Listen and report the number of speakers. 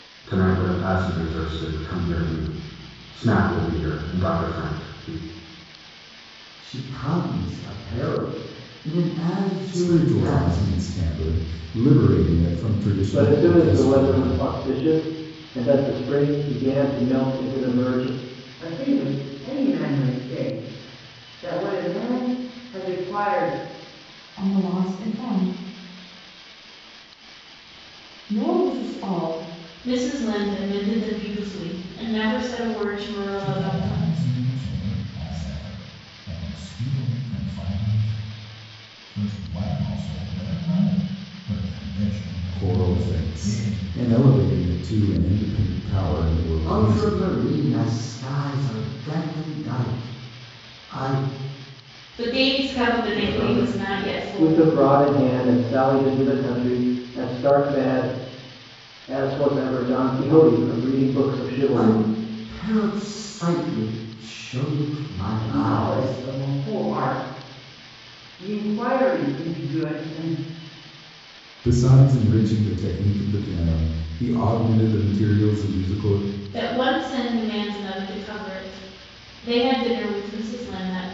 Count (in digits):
8